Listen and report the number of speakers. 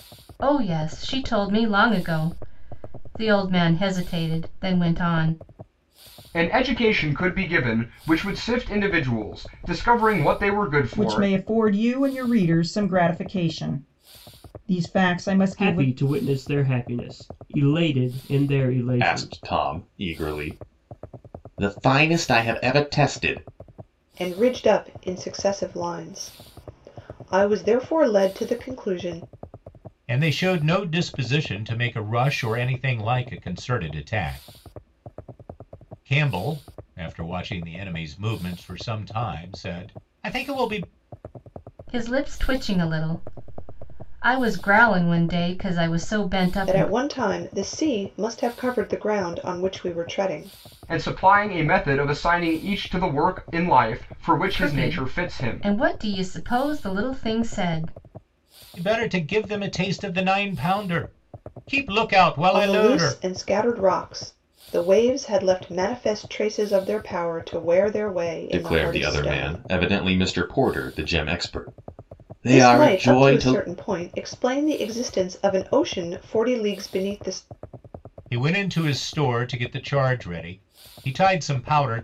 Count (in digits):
7